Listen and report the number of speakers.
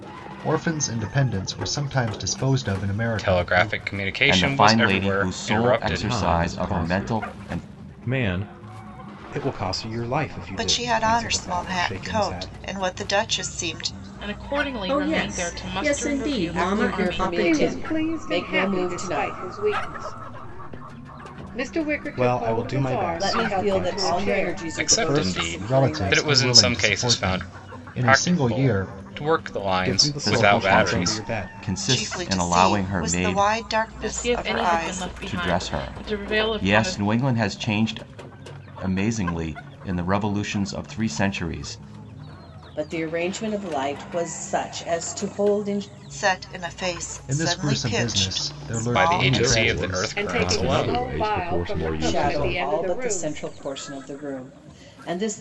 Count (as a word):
ten